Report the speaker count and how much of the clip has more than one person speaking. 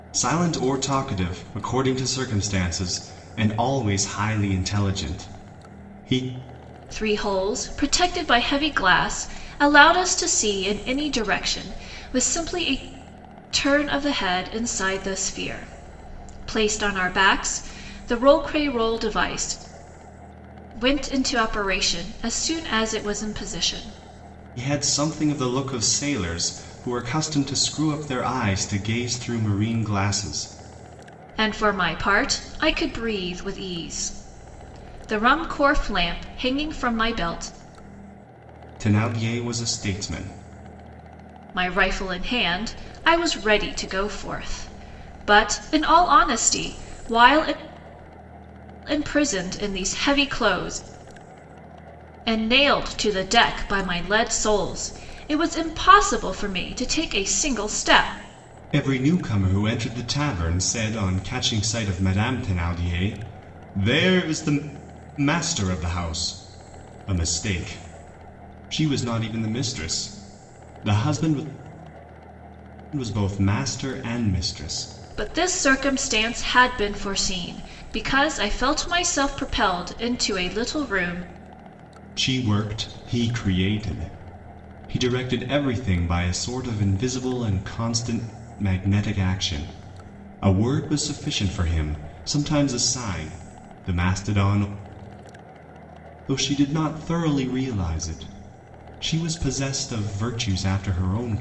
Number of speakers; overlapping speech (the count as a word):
two, no overlap